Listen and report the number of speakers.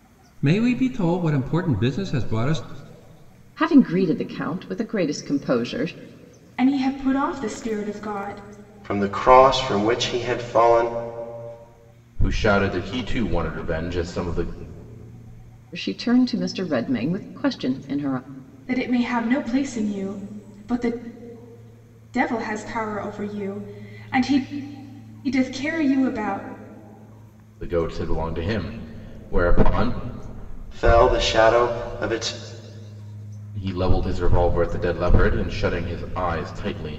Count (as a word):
five